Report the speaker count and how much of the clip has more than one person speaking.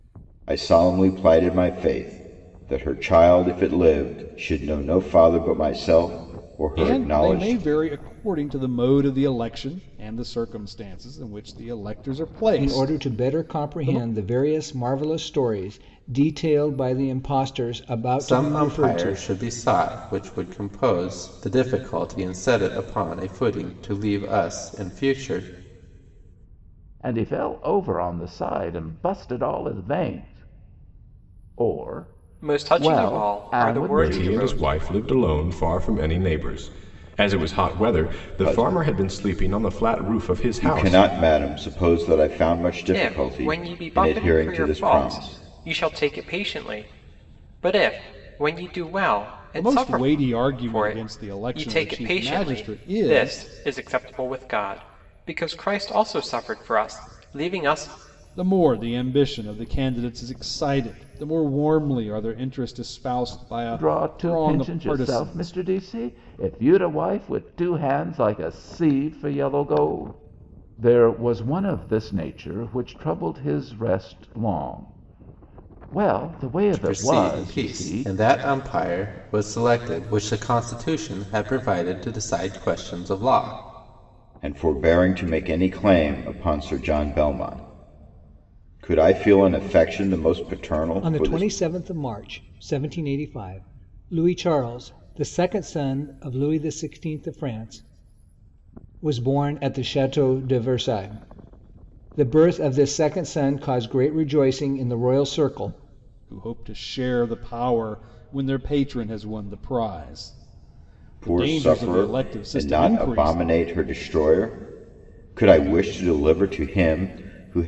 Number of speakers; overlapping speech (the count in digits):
7, about 17%